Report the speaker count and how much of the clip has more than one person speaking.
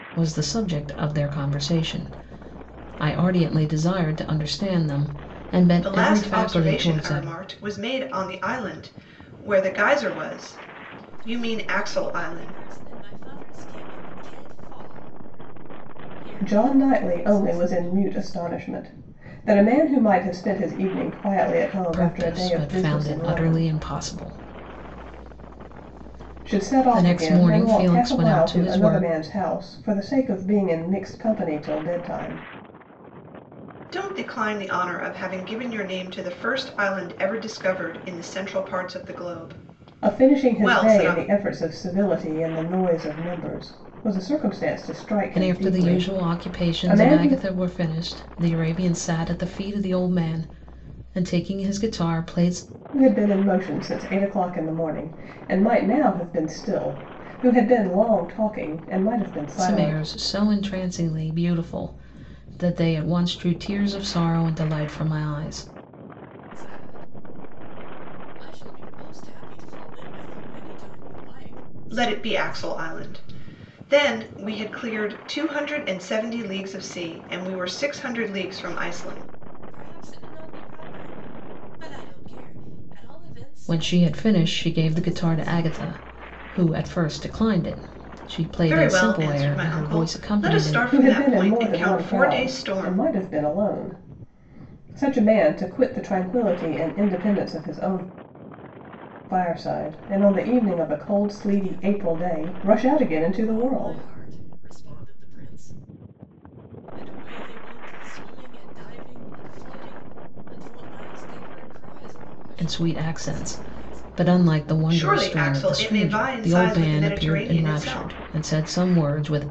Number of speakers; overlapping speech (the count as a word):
four, about 25%